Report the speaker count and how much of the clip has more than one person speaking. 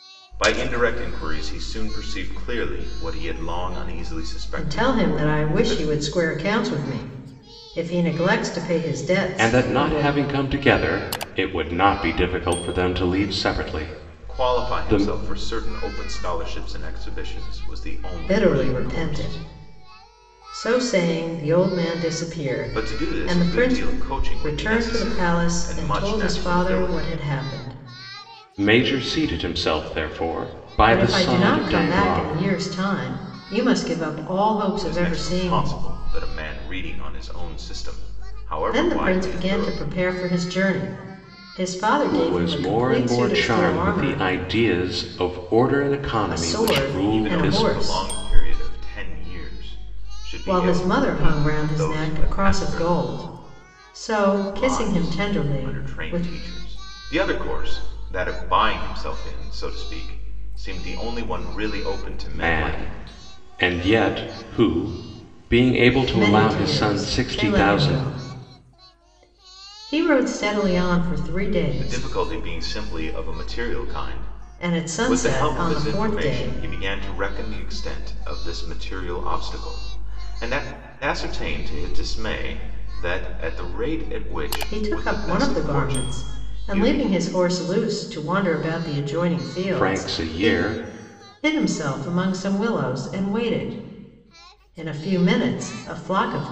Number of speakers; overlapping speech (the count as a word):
three, about 30%